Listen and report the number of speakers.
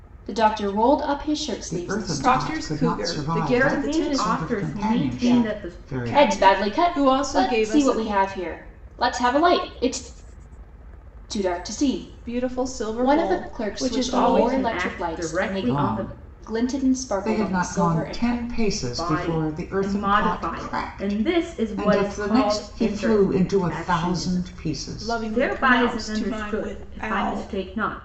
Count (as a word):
four